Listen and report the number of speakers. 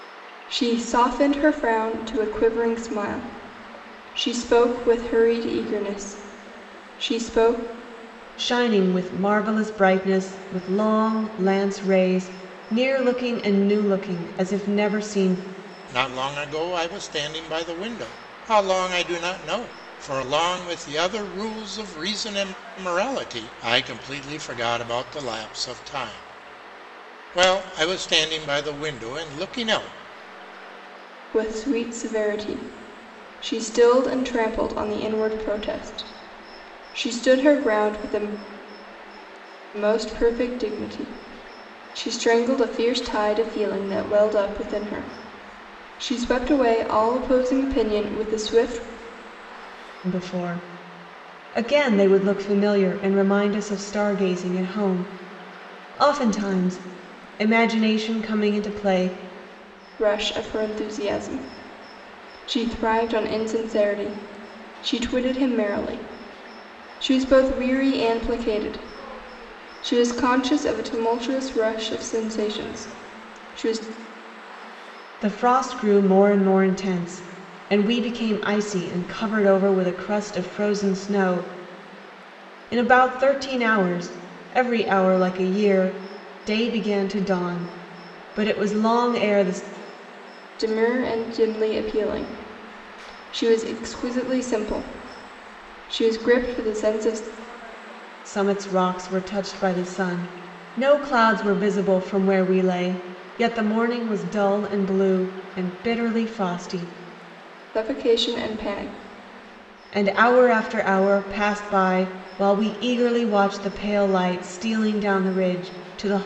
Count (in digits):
3